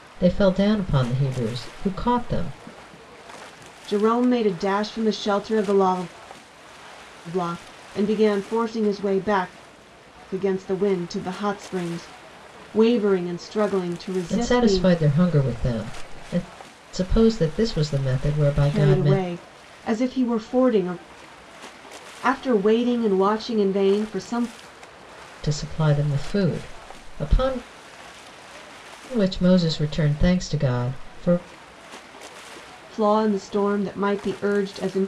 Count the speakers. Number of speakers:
2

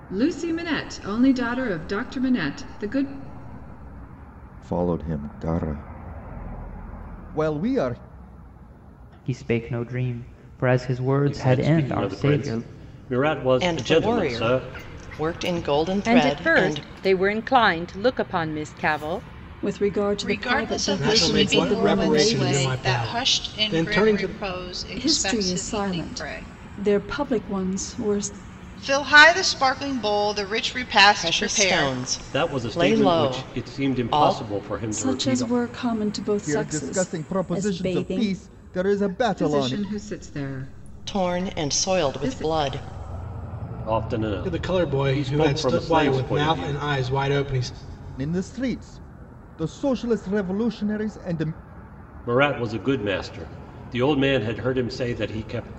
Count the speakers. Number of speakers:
9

